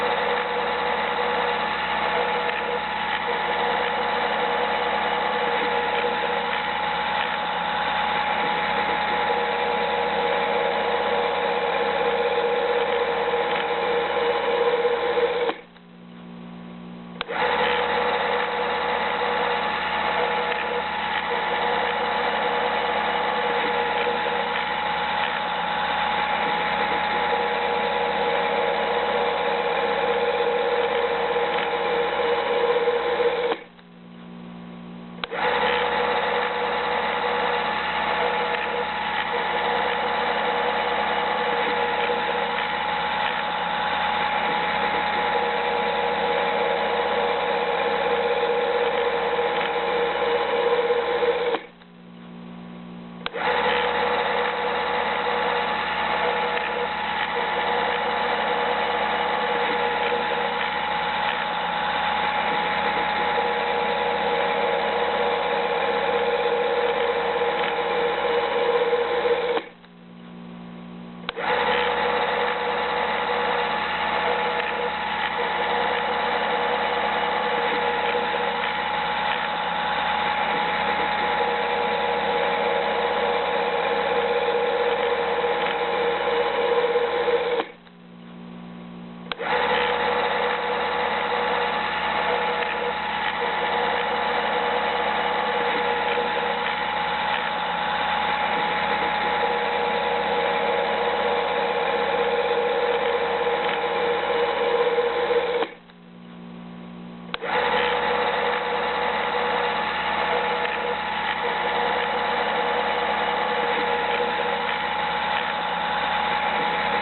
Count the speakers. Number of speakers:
zero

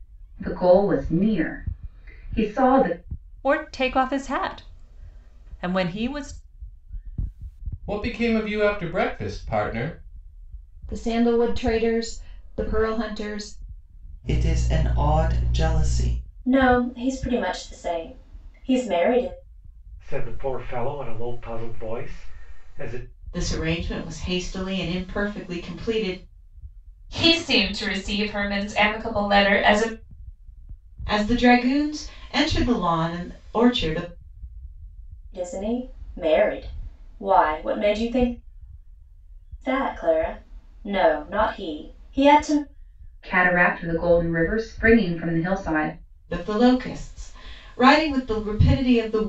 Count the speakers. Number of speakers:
nine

